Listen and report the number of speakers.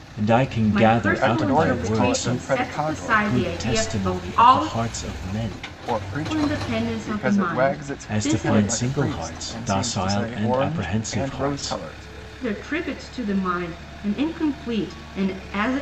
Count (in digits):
3